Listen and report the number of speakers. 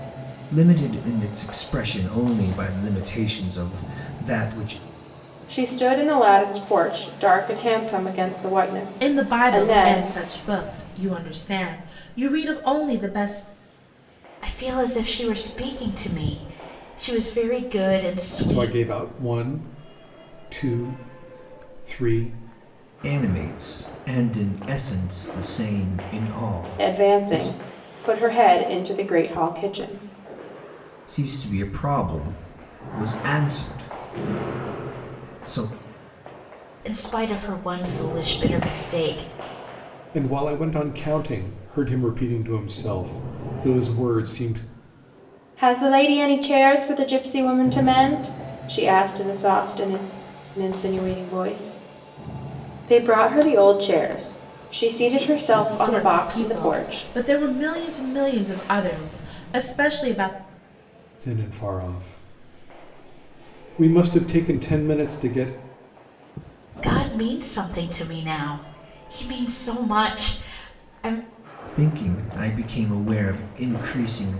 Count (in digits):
5